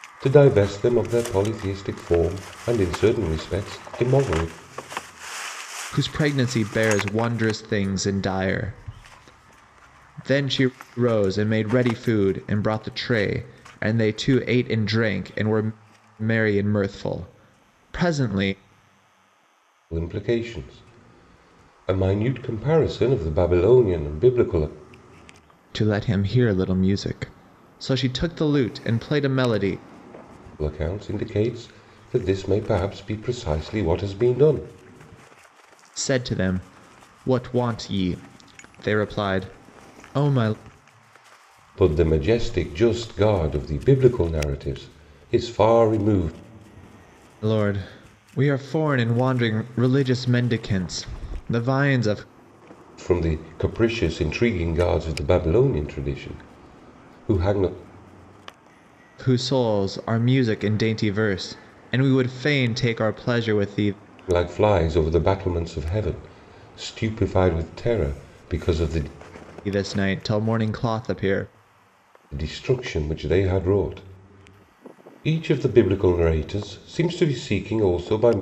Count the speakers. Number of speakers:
two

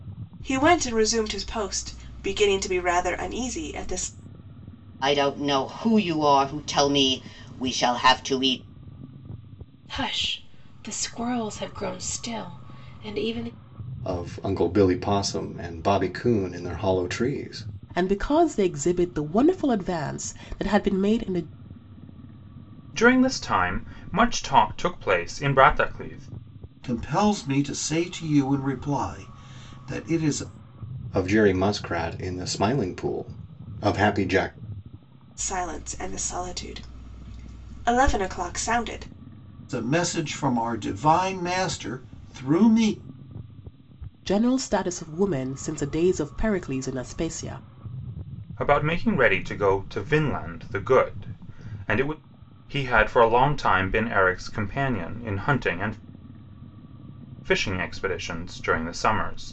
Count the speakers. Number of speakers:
seven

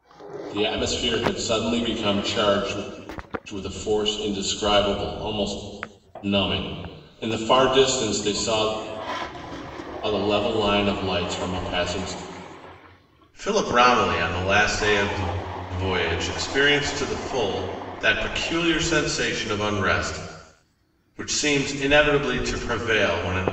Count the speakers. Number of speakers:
one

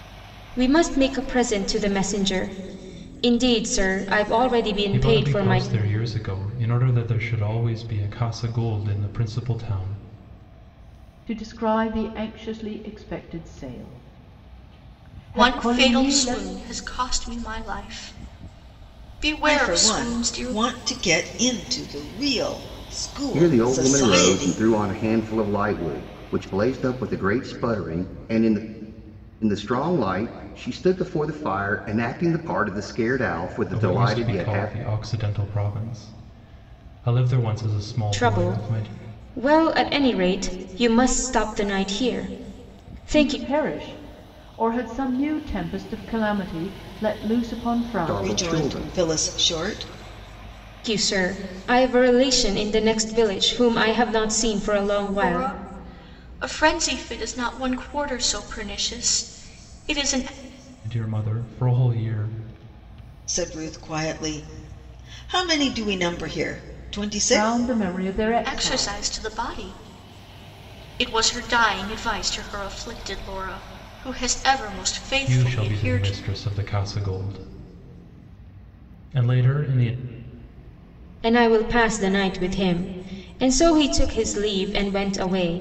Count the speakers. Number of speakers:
six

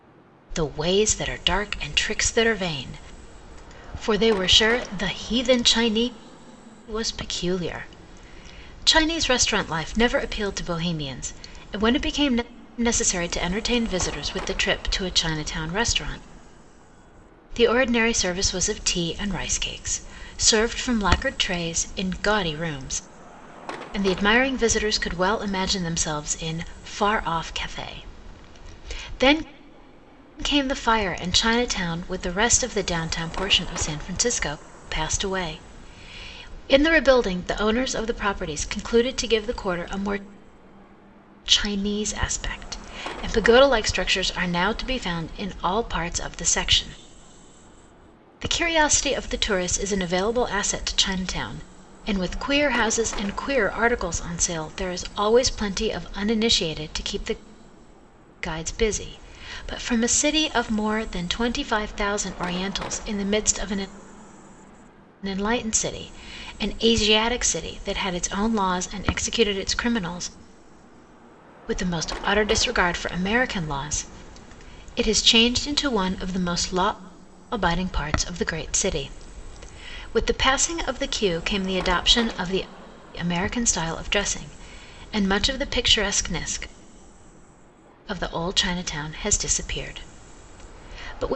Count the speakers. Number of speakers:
one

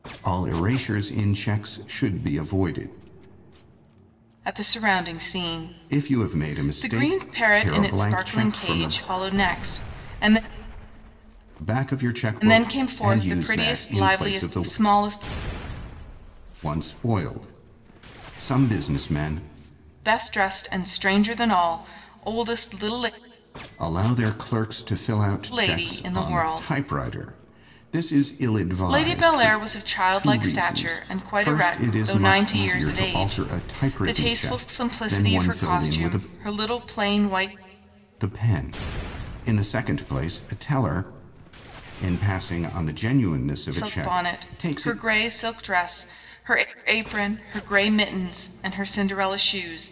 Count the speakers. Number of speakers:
two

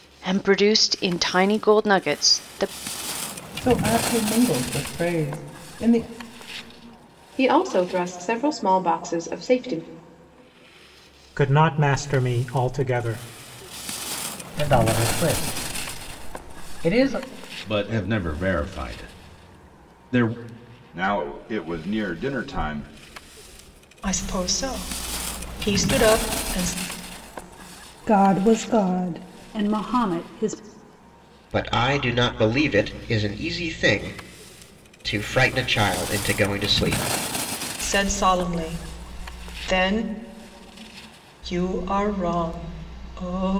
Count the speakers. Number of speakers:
ten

